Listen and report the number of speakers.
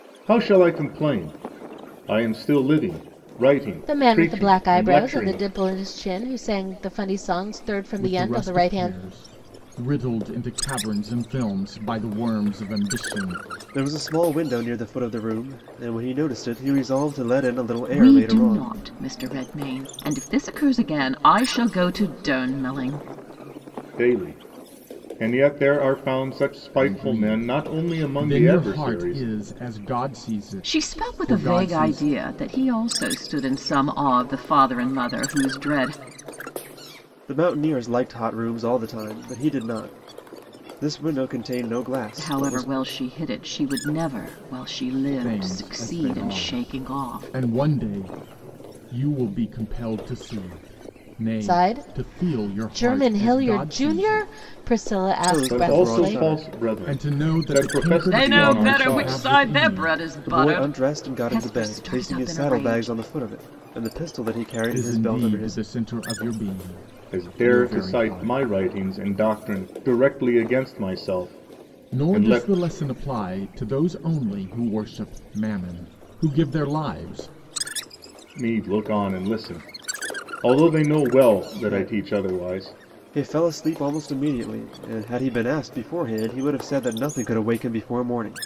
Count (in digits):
5